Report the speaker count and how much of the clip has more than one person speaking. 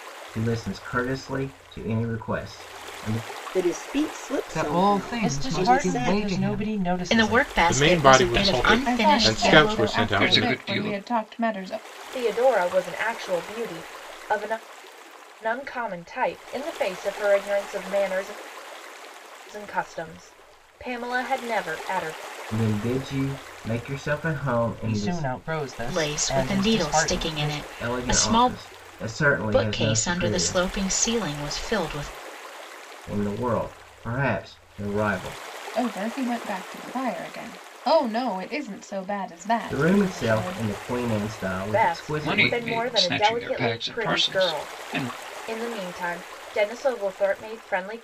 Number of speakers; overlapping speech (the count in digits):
9, about 31%